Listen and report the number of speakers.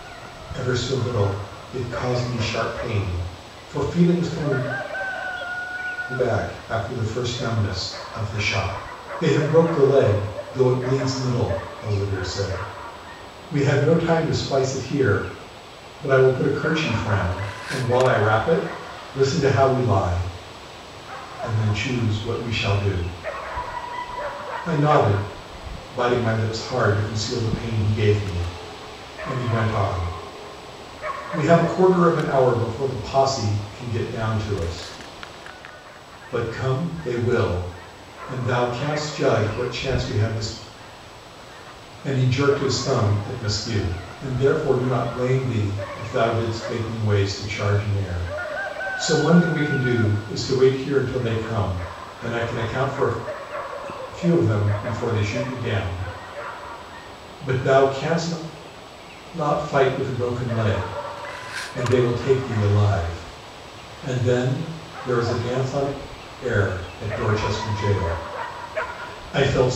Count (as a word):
one